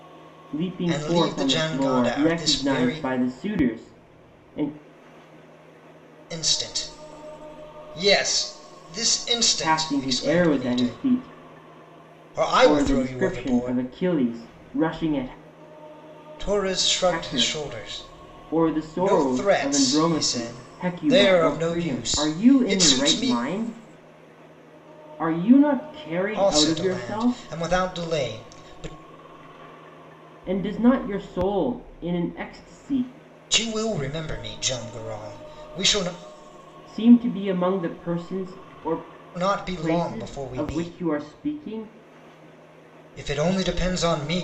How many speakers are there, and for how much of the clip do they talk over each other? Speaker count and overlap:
2, about 28%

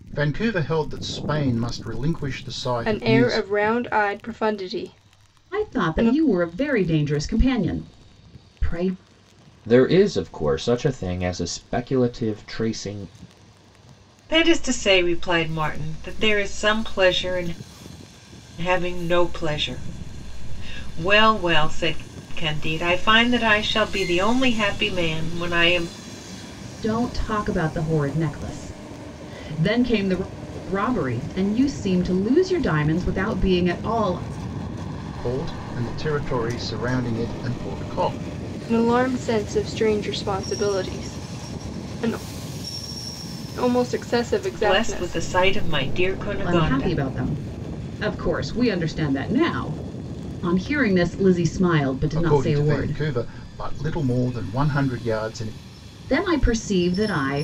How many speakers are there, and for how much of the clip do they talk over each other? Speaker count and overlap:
5, about 6%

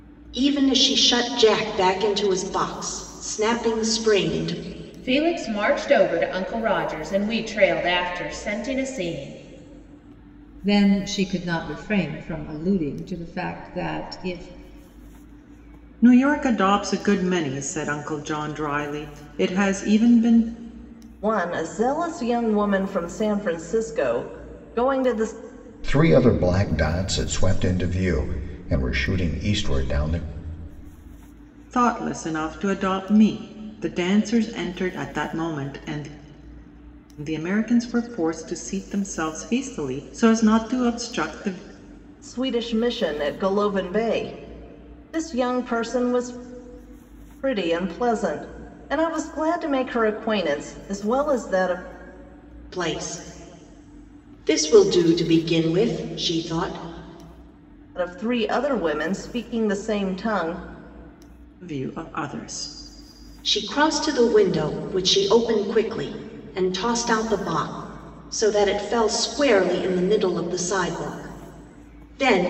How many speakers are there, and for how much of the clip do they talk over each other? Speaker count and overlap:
6, no overlap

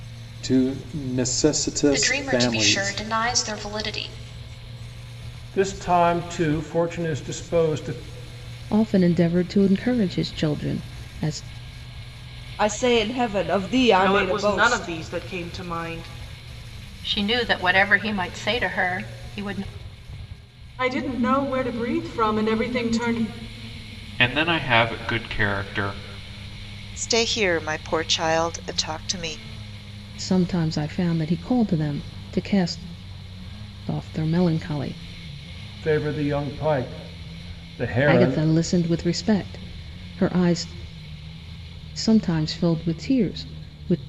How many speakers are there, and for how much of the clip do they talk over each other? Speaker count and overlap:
10, about 6%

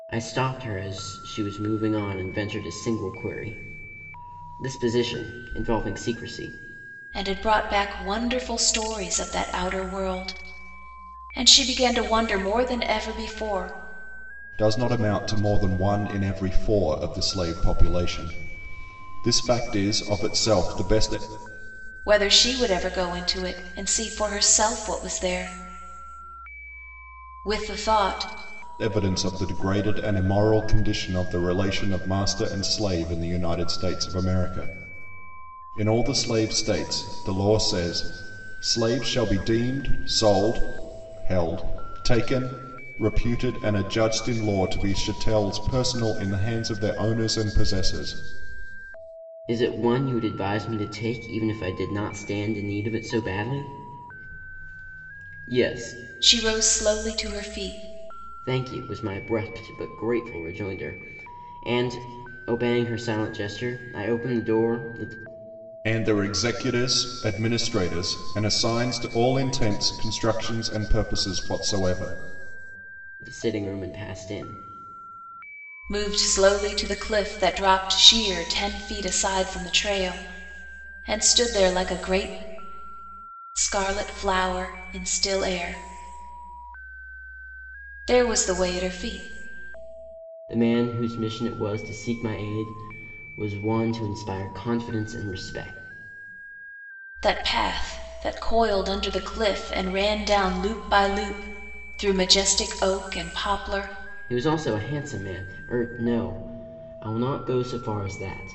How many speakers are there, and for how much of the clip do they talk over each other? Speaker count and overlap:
3, no overlap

